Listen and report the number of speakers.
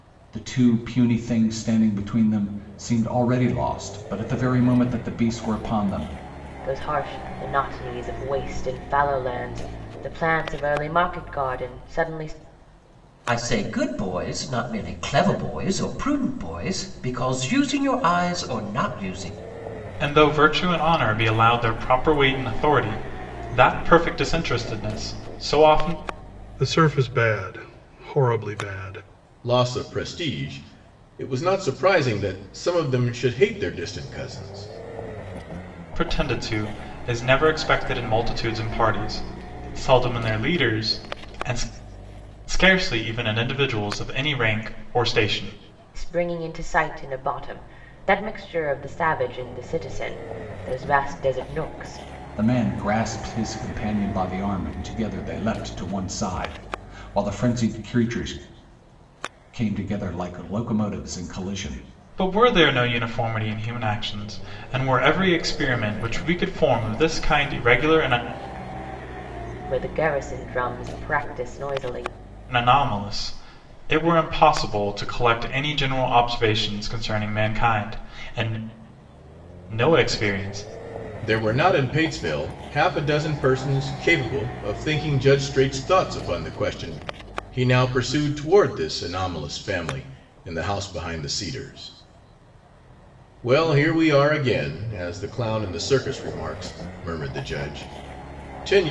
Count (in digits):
6